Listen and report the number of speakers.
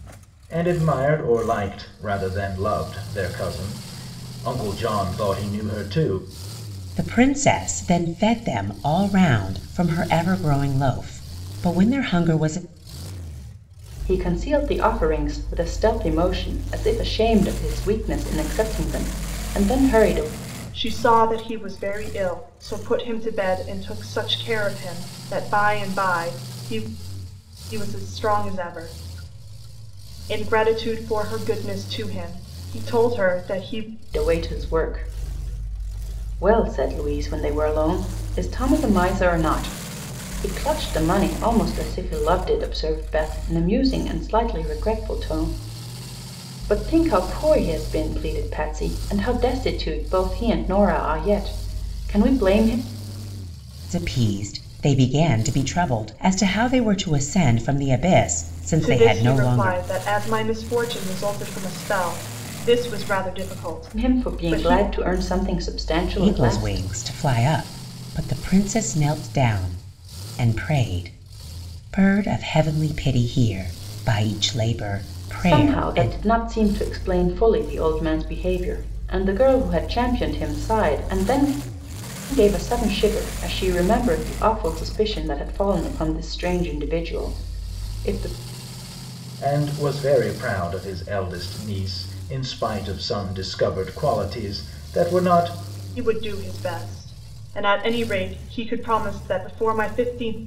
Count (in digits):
4